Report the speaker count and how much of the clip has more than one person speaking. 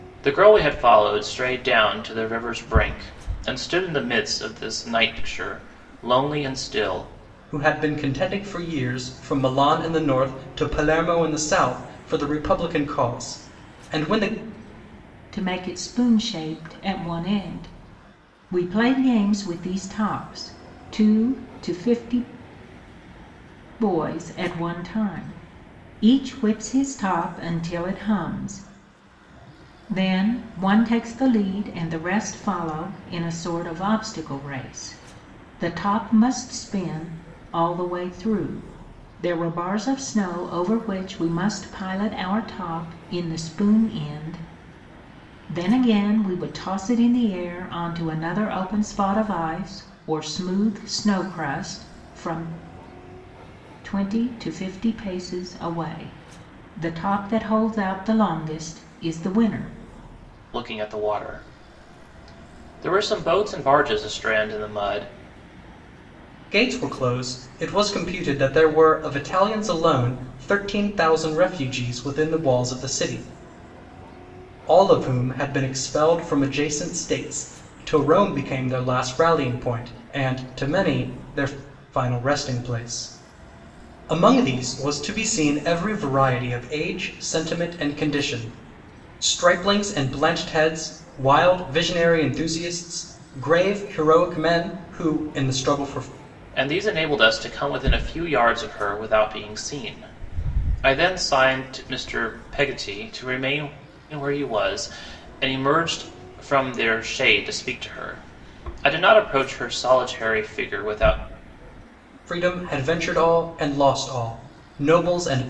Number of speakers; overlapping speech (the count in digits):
3, no overlap